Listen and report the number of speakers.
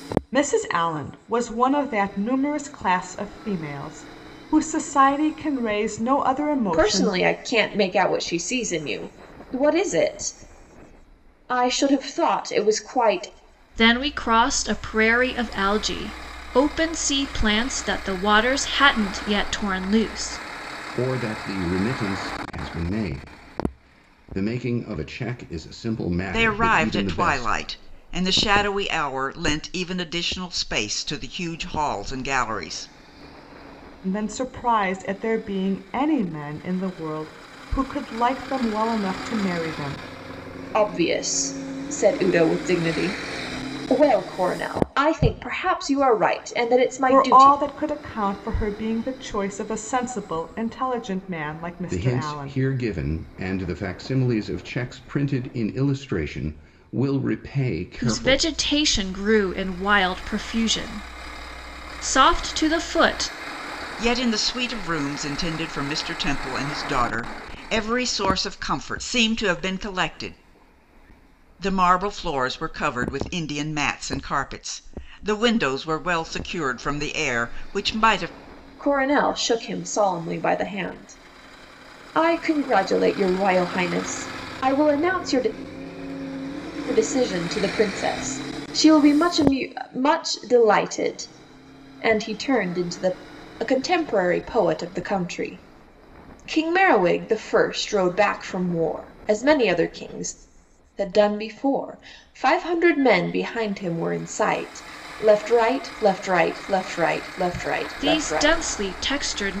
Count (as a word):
five